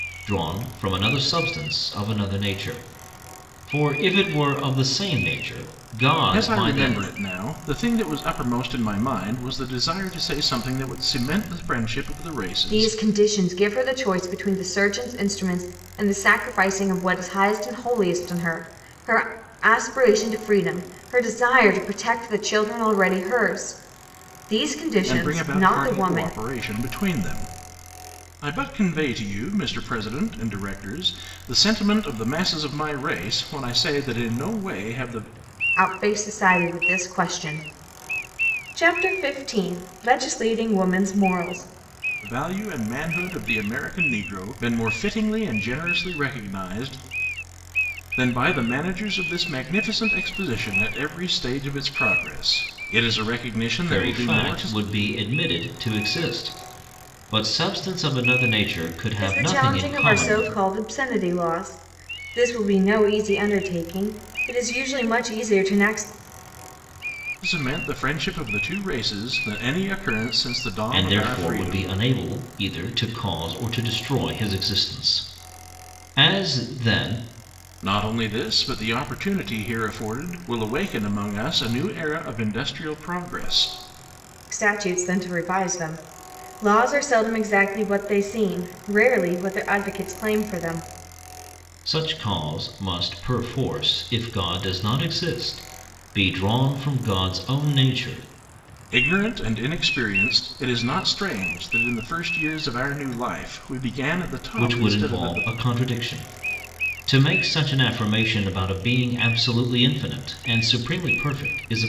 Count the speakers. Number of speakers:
three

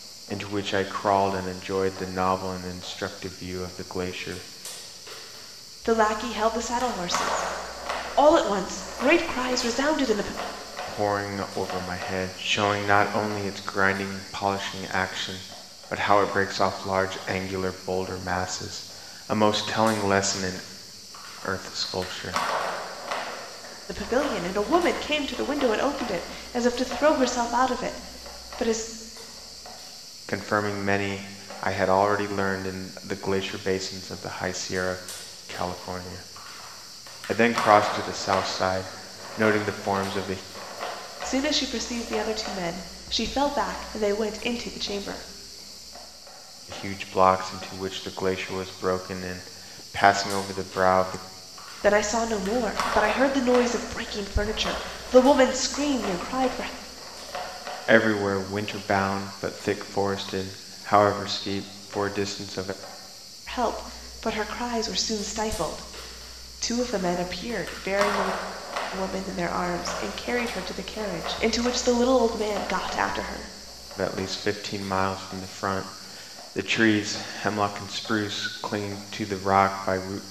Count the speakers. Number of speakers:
two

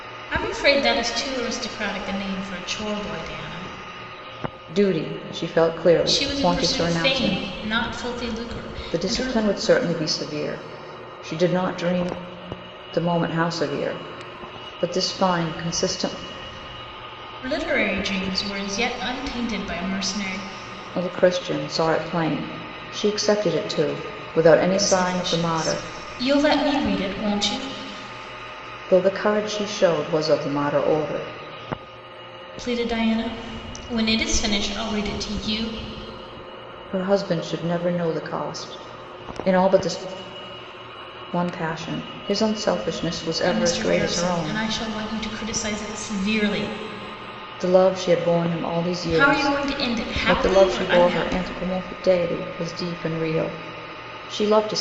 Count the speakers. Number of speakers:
two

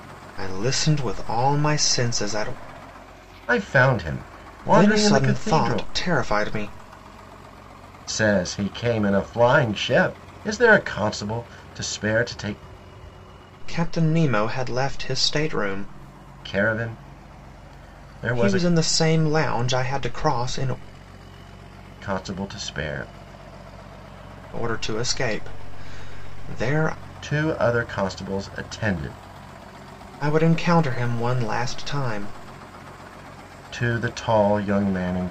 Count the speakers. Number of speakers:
two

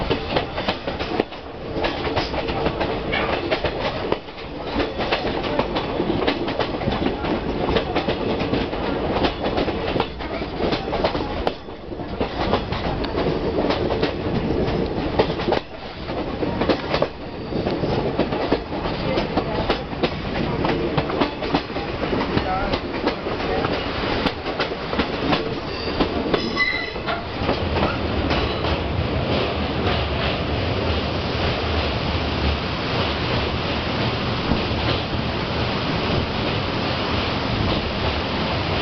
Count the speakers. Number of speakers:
zero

